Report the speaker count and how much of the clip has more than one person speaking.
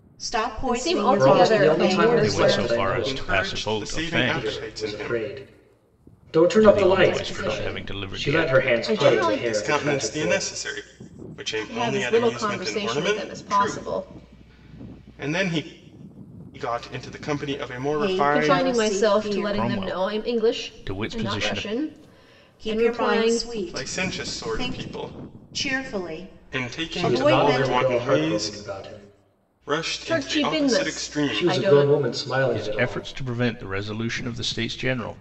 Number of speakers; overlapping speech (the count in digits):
5, about 59%